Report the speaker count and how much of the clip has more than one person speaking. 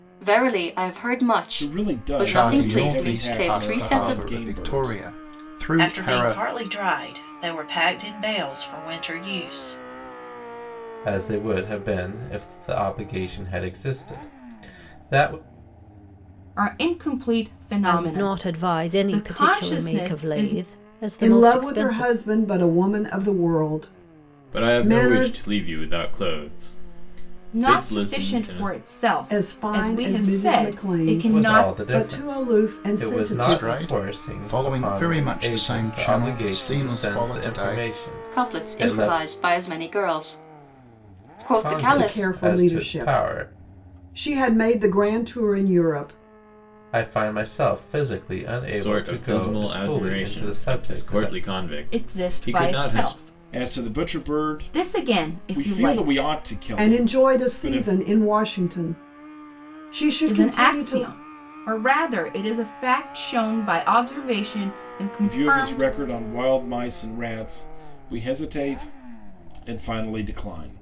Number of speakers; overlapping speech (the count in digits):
9, about 43%